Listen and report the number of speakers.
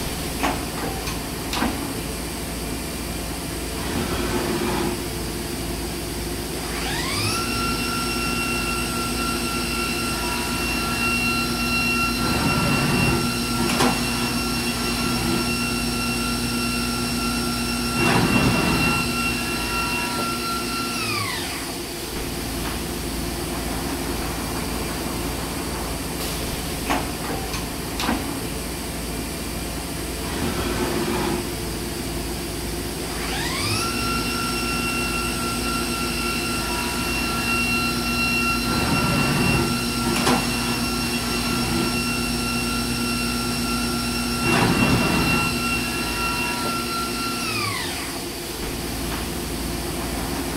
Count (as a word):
zero